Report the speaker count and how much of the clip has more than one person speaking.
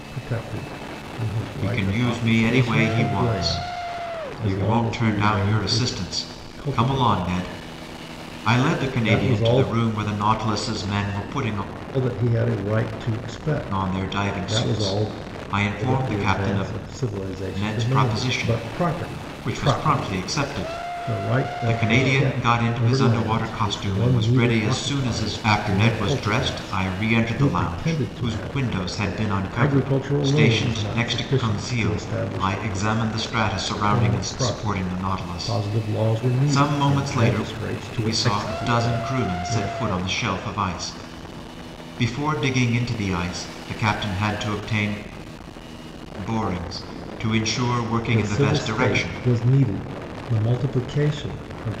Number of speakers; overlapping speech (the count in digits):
2, about 56%